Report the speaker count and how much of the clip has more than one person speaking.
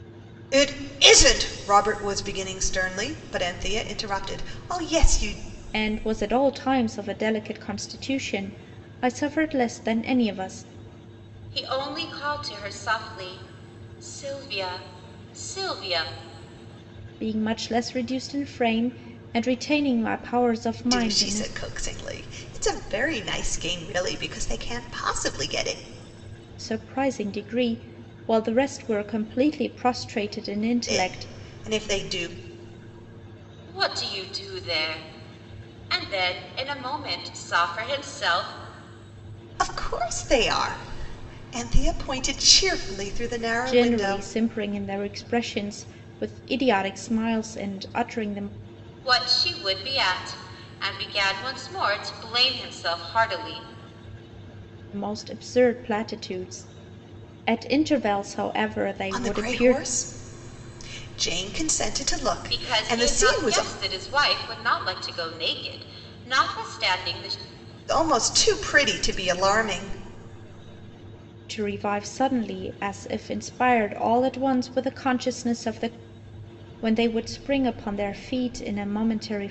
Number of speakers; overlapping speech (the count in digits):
3, about 5%